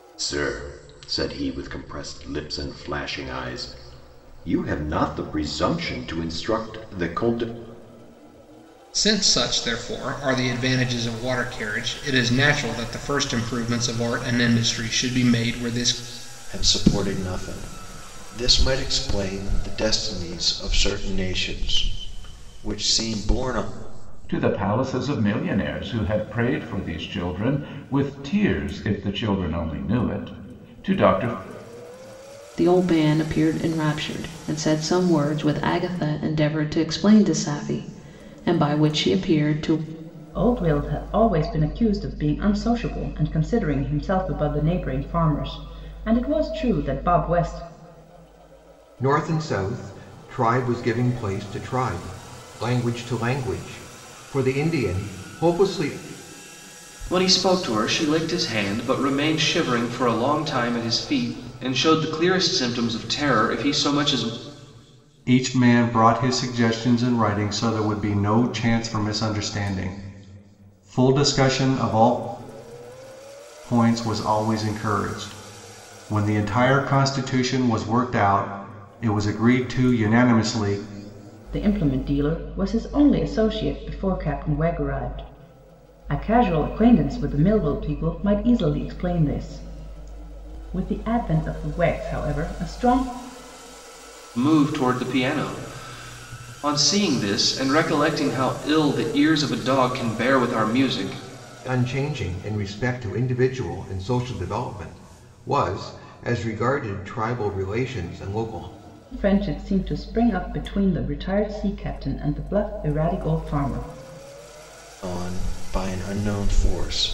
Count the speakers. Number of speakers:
nine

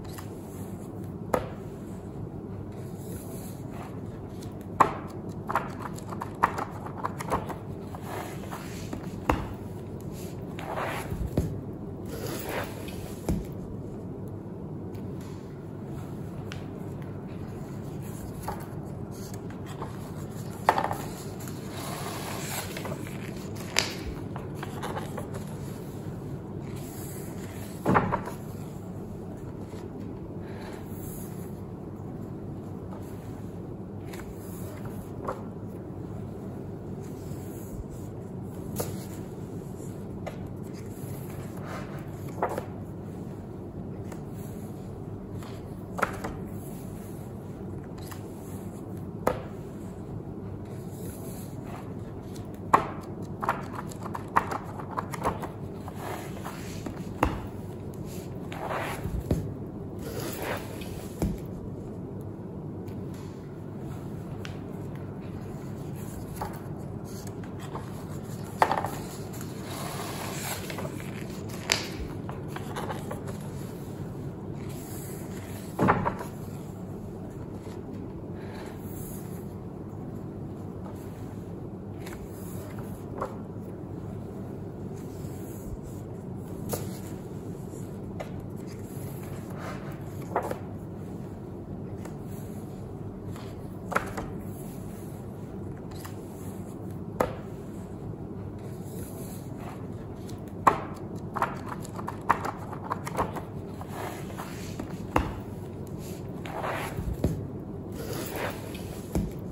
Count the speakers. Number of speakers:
zero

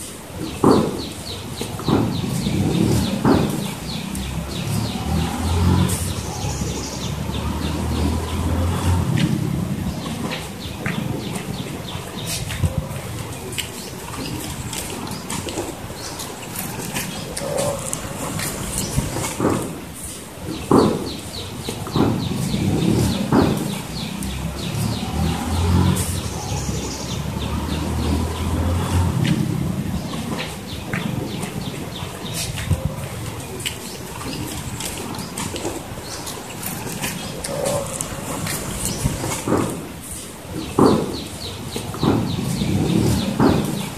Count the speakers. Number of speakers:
zero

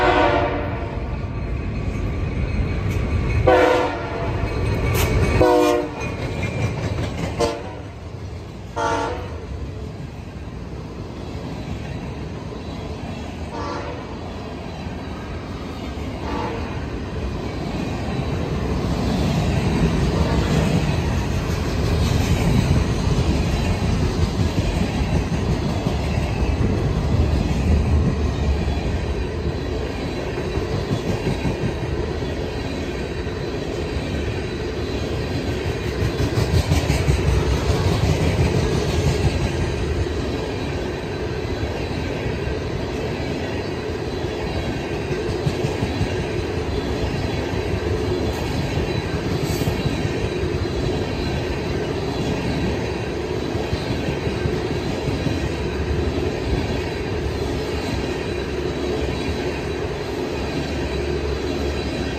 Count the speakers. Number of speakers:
zero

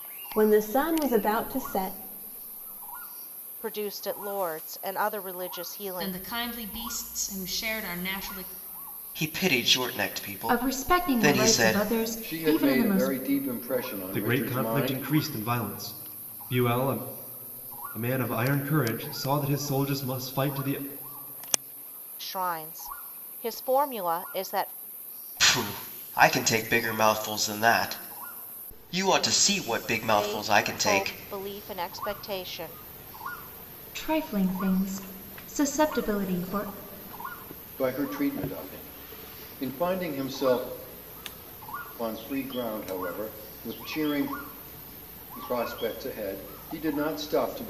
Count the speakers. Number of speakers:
seven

